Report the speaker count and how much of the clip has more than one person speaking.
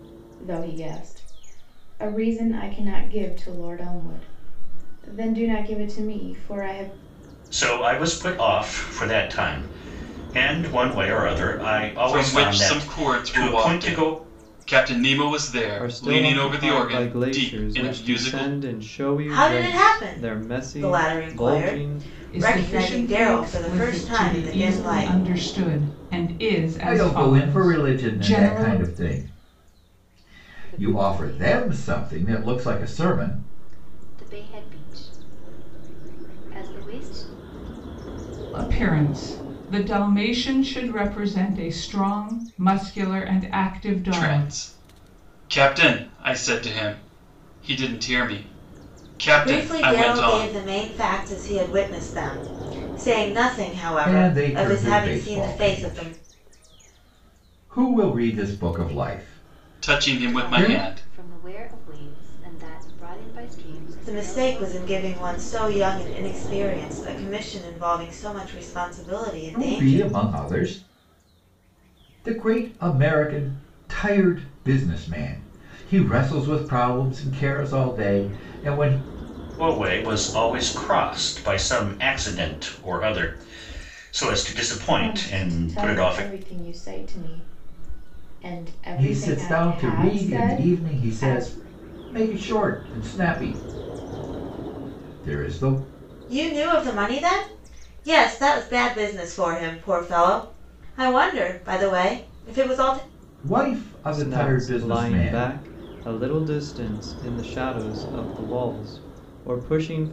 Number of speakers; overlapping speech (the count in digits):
8, about 27%